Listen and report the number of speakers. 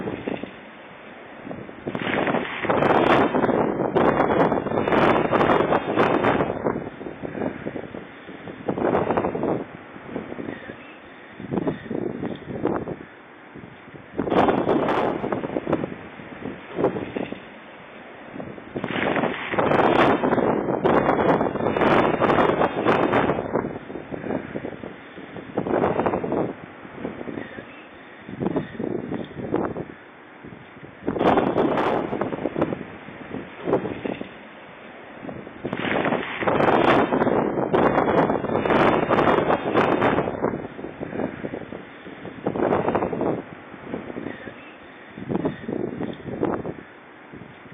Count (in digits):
0